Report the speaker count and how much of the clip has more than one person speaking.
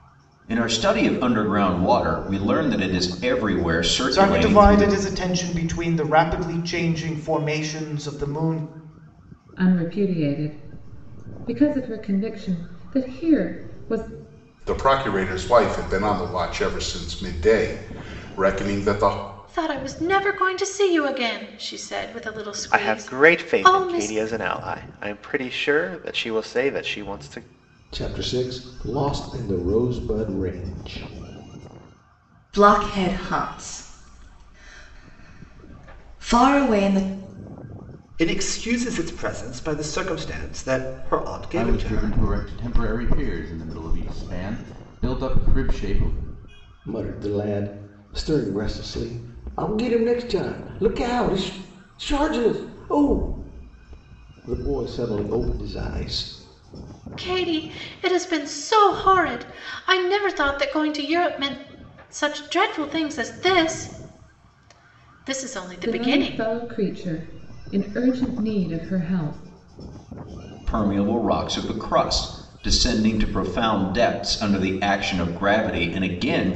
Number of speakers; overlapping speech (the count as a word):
ten, about 5%